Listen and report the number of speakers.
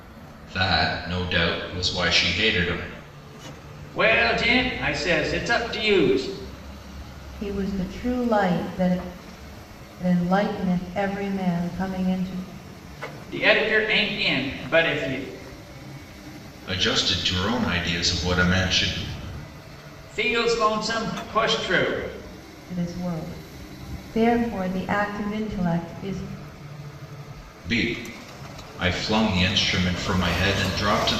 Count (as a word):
three